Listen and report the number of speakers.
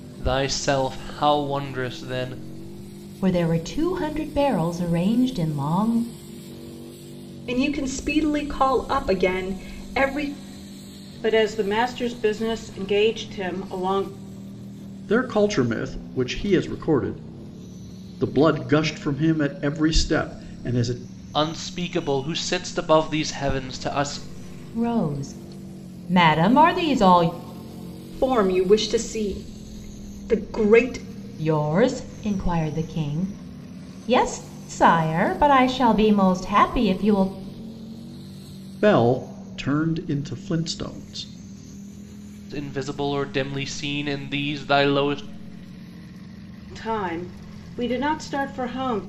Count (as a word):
five